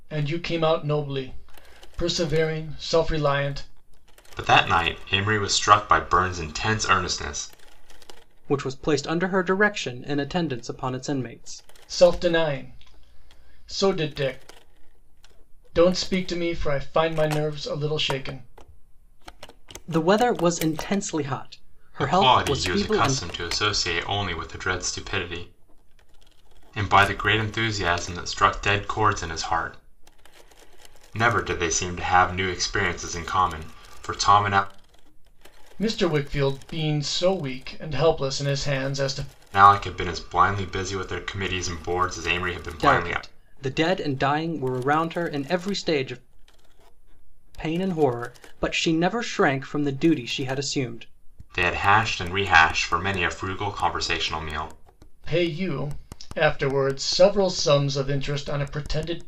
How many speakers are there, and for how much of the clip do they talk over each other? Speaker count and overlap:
three, about 3%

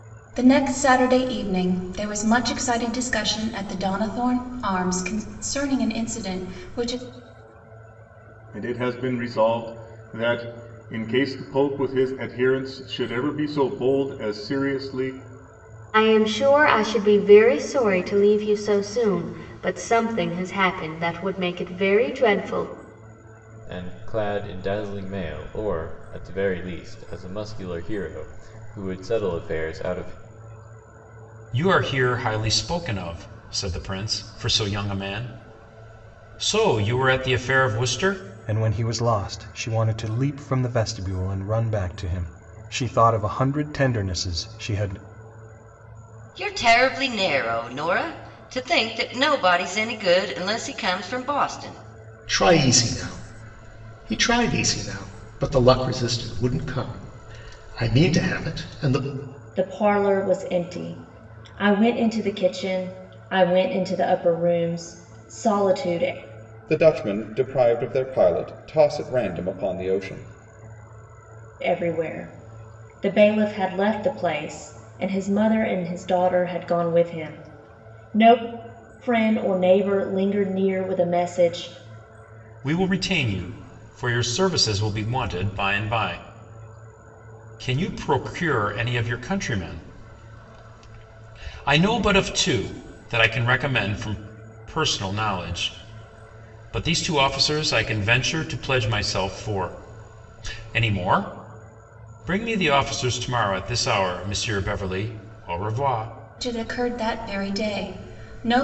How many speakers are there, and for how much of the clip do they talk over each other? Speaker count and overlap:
ten, no overlap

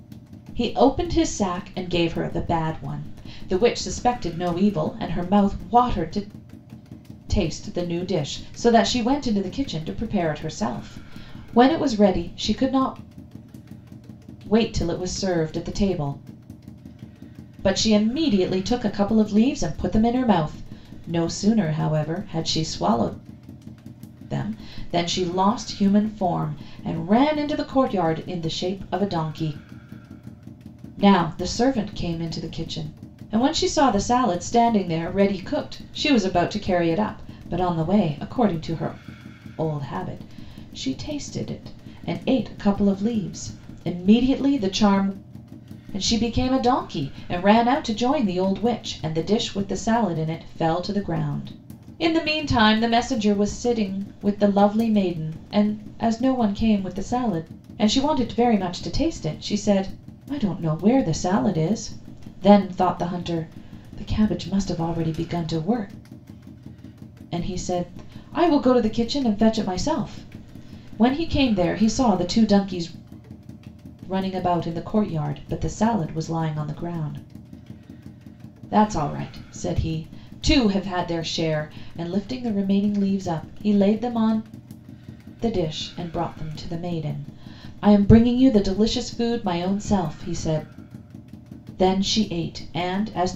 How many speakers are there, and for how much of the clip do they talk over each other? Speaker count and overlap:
one, no overlap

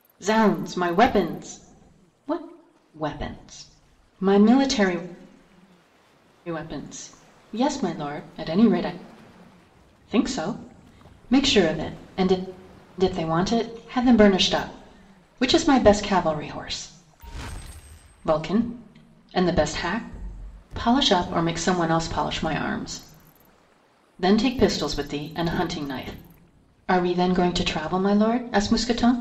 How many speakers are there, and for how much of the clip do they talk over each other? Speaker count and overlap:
one, no overlap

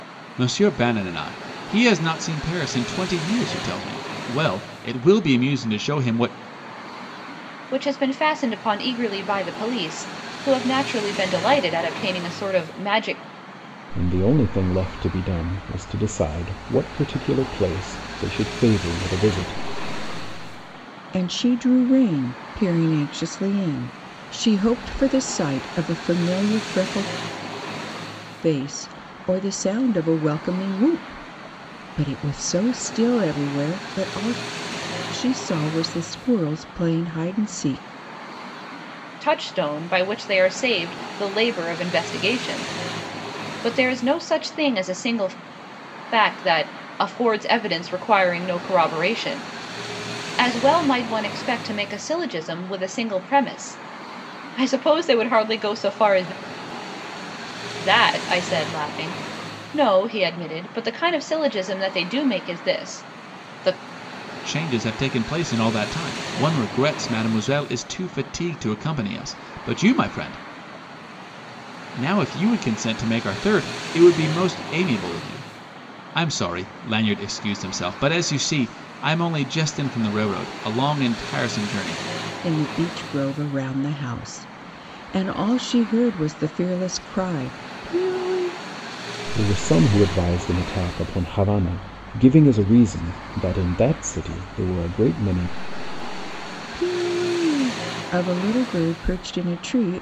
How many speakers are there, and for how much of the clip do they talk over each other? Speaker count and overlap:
four, no overlap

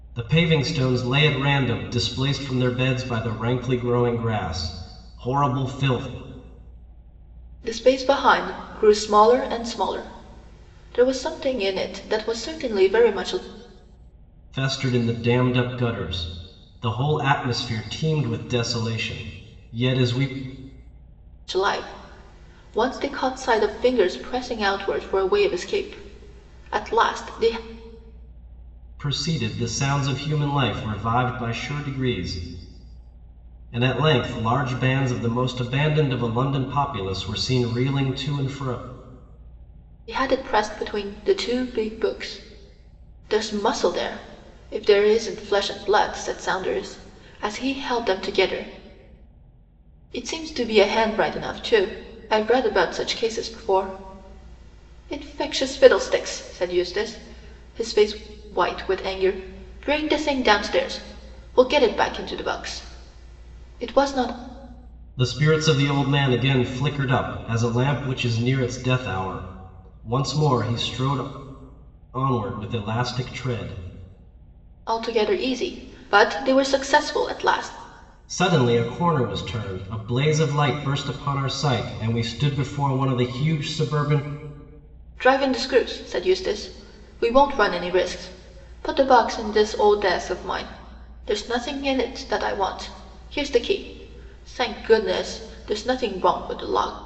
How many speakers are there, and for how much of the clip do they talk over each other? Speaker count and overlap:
two, no overlap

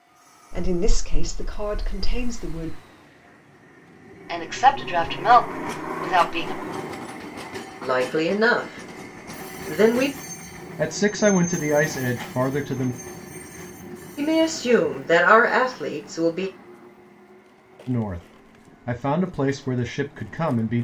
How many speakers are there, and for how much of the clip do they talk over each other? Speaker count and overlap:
four, no overlap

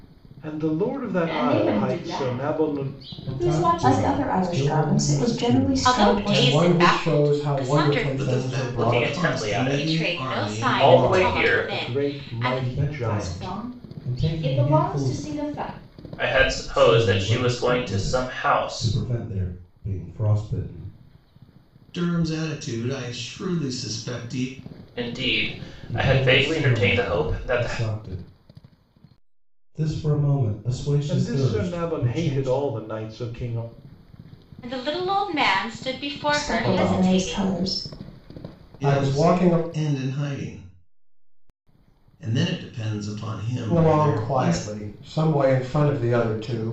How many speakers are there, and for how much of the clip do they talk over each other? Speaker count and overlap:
eight, about 49%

